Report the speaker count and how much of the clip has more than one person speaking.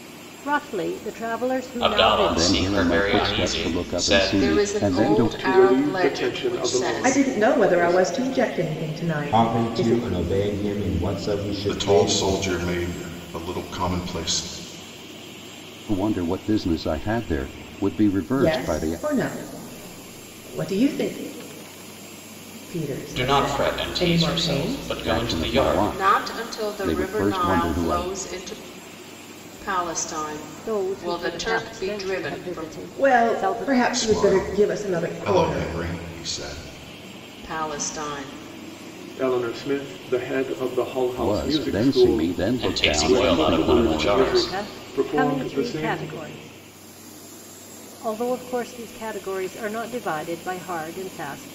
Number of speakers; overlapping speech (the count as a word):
eight, about 45%